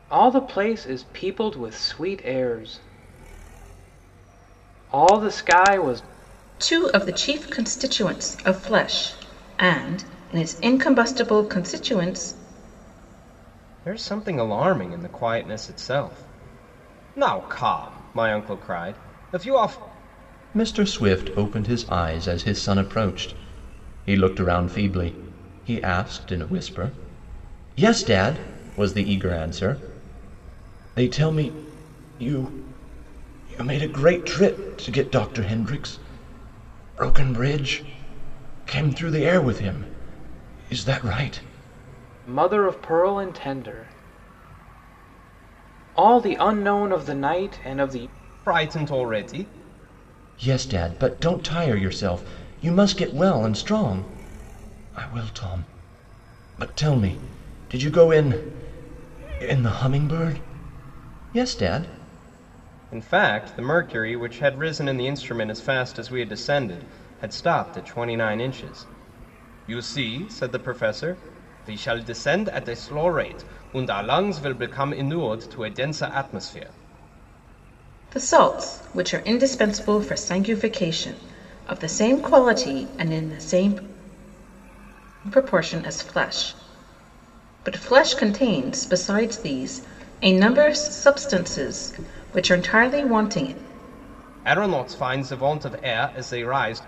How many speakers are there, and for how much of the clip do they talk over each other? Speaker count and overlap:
4, no overlap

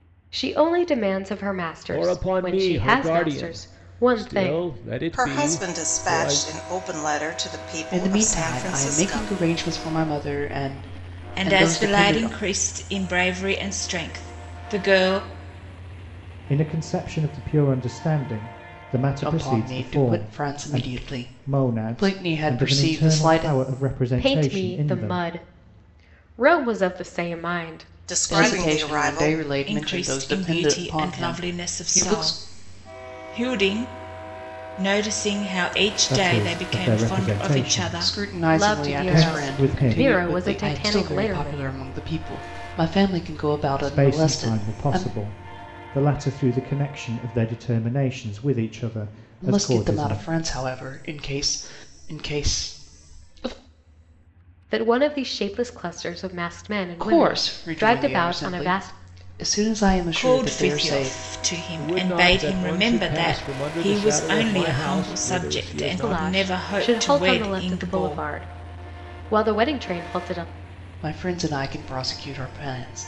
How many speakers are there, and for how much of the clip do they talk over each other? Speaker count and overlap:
6, about 45%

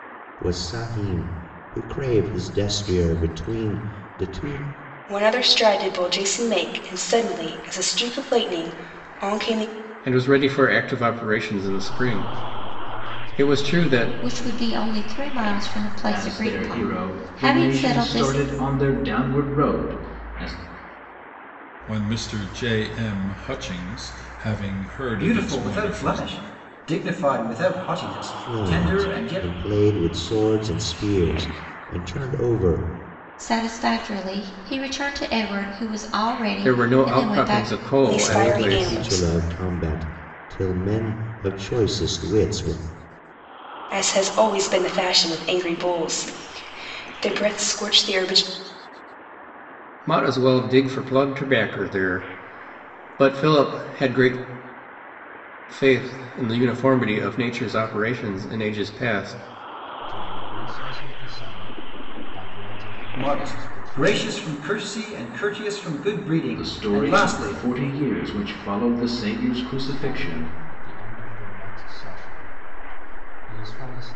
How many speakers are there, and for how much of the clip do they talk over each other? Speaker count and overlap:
8, about 19%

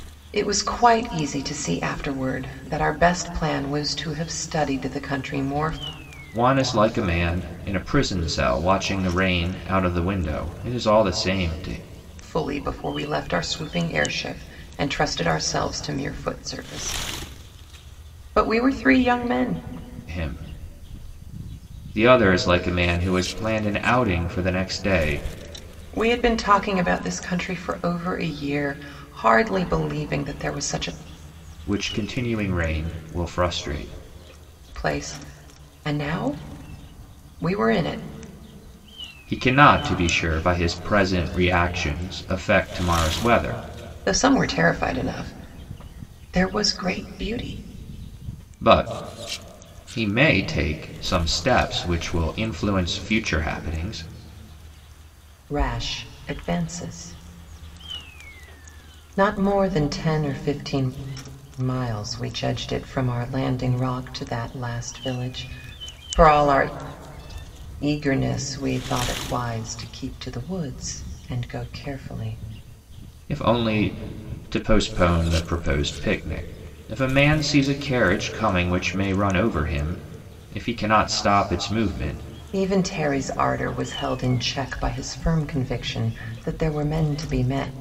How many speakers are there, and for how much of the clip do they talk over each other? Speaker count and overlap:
2, no overlap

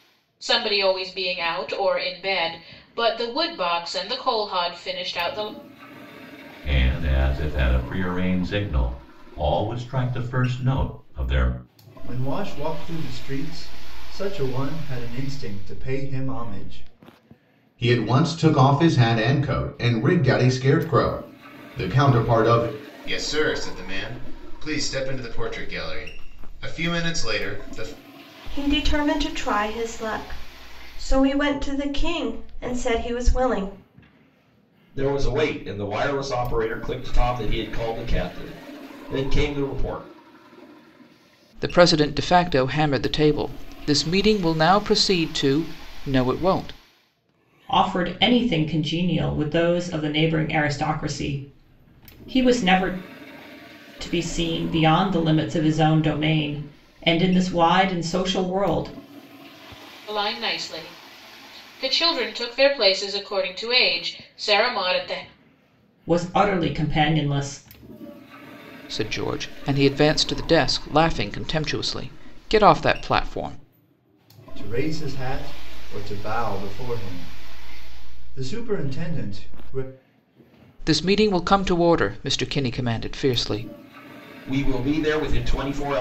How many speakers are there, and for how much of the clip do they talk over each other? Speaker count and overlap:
9, no overlap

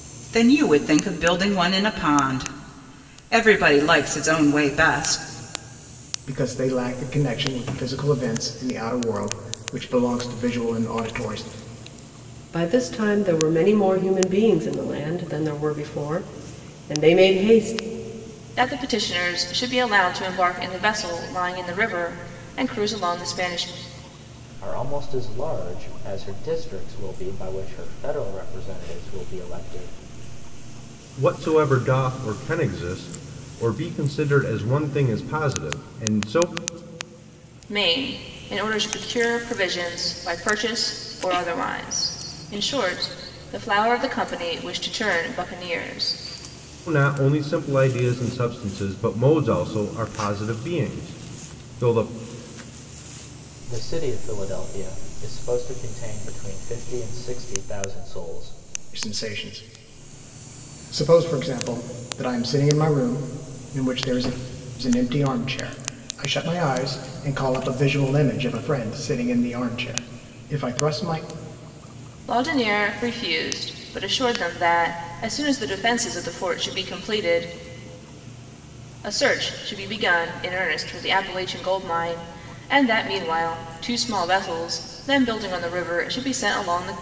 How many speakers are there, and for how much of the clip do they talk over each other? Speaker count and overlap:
6, no overlap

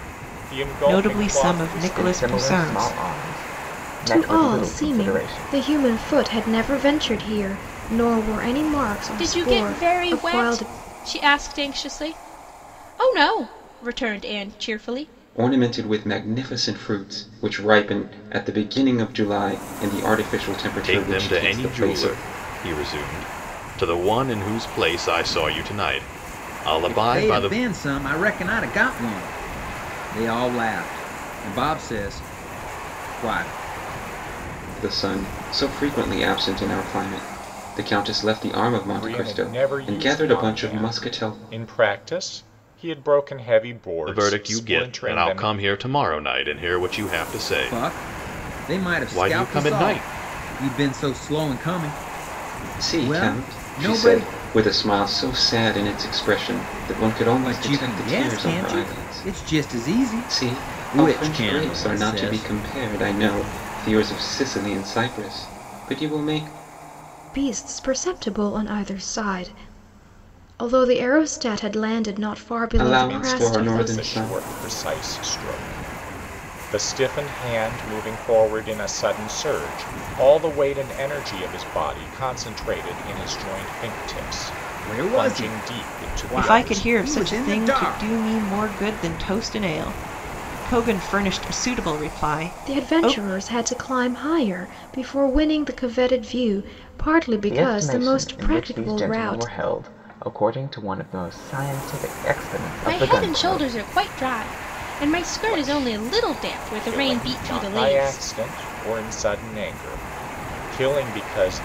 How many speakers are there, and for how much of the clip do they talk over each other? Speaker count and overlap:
8, about 28%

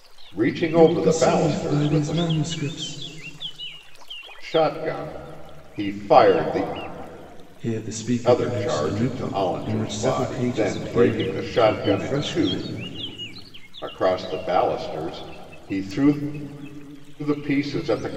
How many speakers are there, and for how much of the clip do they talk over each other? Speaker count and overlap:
2, about 31%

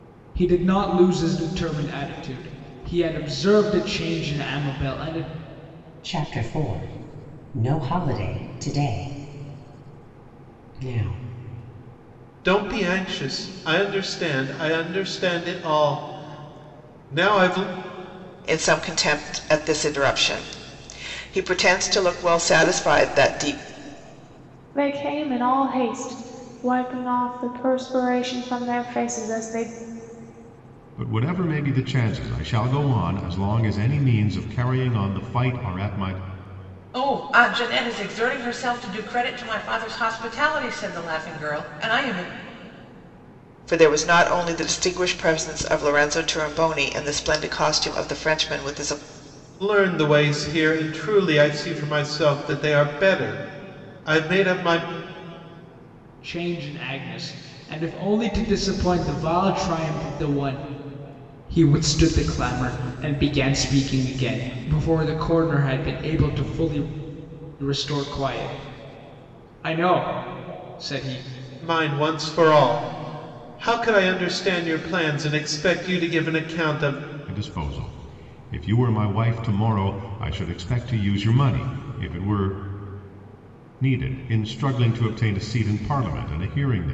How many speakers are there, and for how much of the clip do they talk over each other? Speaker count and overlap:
7, no overlap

